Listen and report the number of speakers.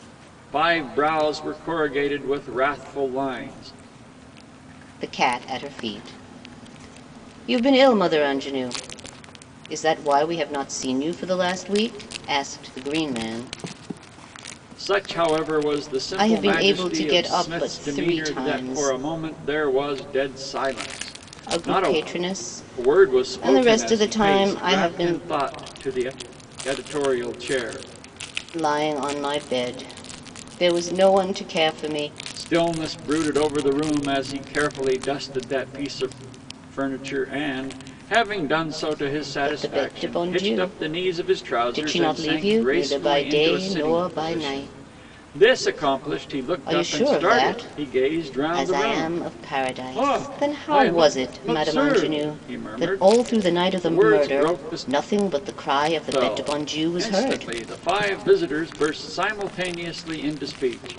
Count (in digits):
2